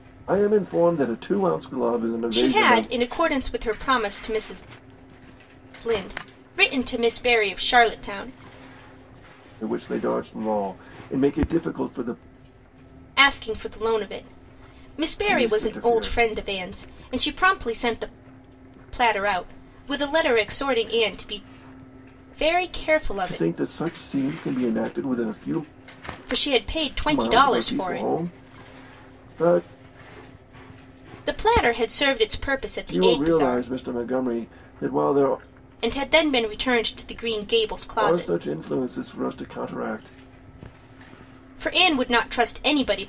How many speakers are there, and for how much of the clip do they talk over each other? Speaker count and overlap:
two, about 10%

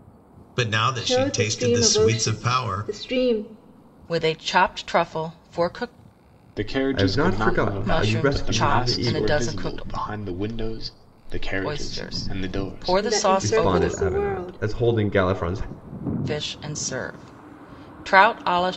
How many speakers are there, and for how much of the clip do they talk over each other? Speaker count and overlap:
five, about 42%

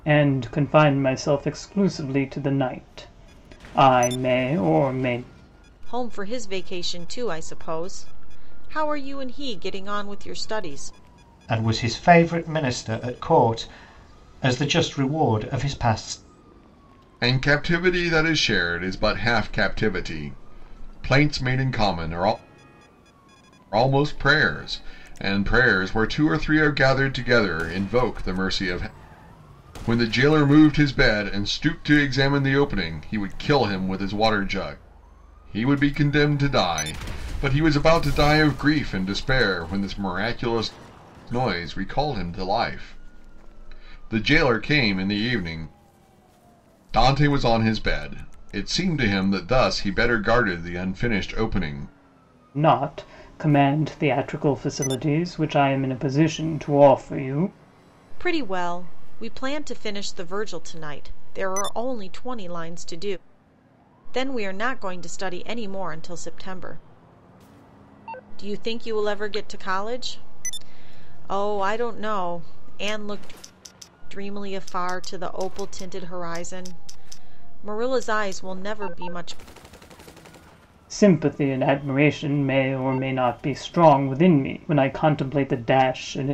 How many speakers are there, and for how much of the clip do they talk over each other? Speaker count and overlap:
four, no overlap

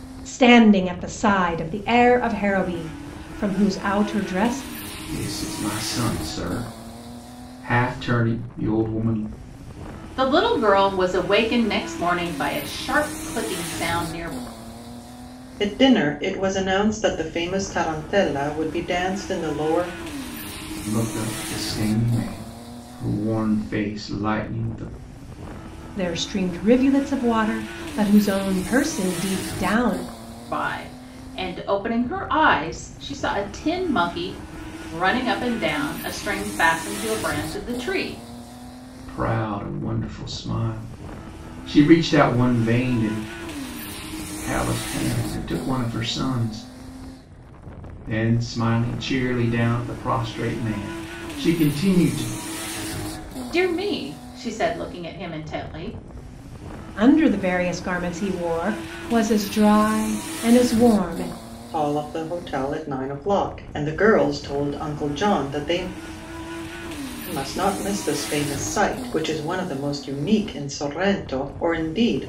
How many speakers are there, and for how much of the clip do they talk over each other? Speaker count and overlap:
four, no overlap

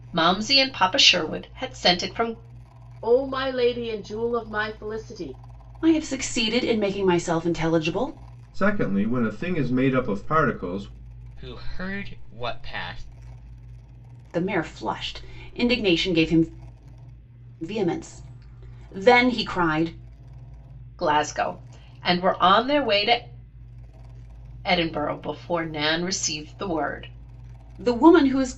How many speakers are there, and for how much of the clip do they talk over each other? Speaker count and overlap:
five, no overlap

